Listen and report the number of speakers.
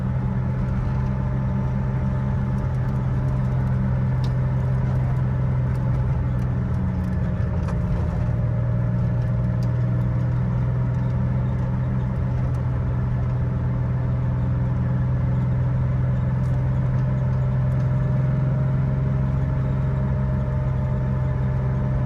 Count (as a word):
zero